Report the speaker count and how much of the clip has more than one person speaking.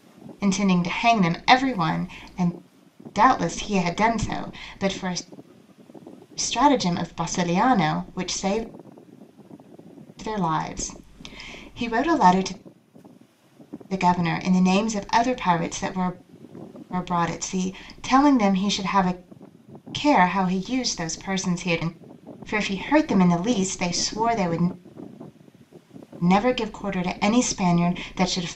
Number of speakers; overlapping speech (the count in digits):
1, no overlap